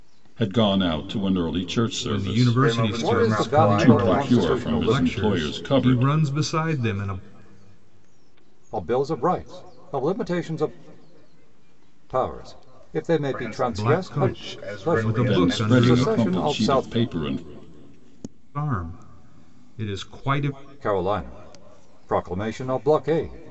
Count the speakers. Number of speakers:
4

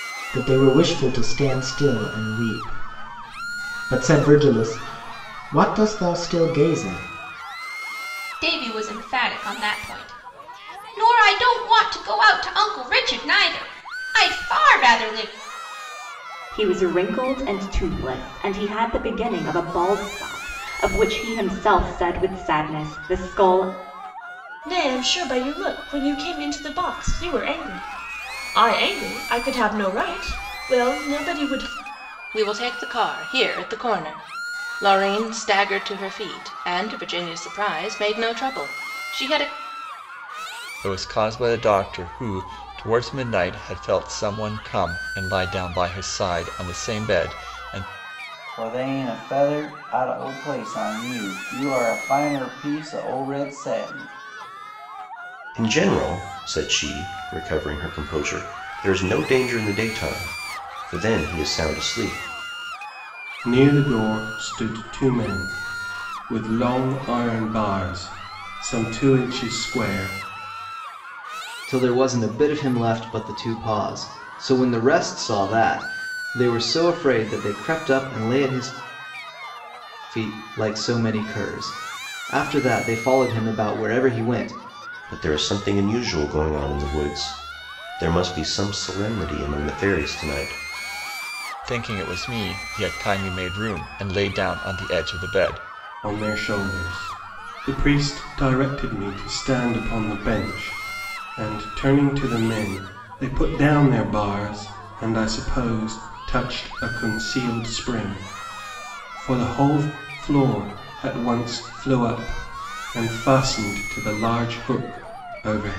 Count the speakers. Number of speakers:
10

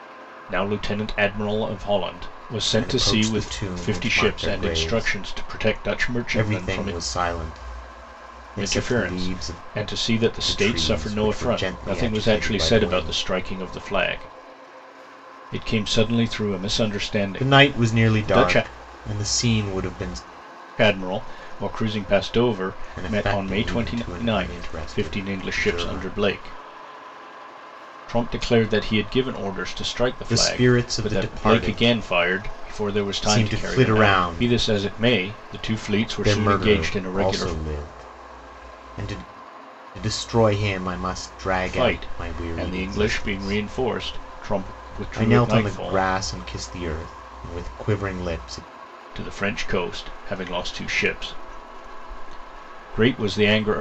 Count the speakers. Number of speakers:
2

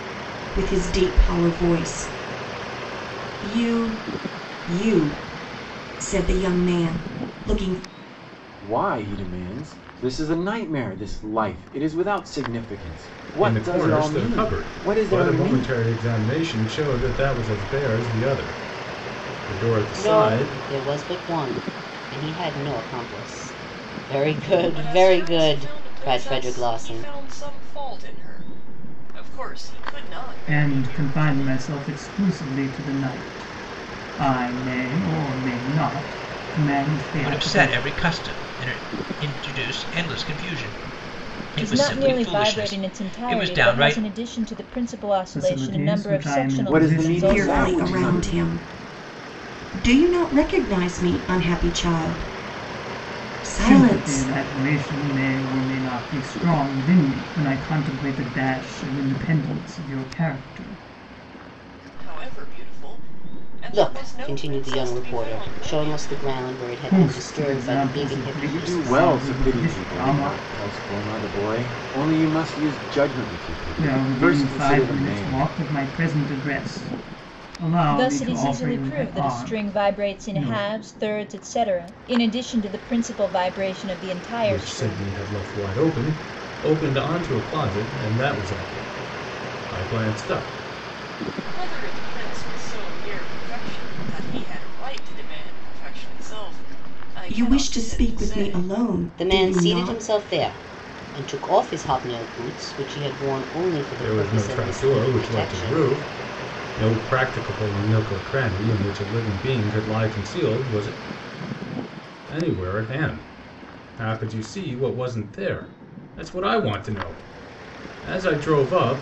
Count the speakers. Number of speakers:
8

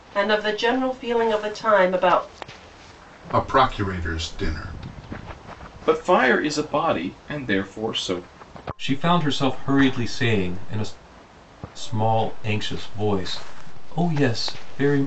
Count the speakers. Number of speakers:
4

